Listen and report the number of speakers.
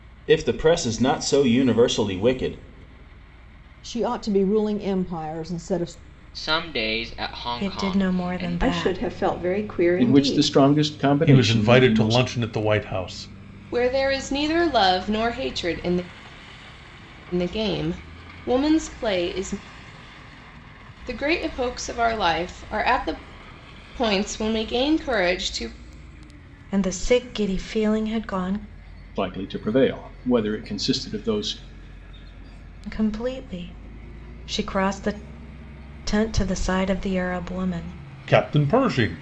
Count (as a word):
eight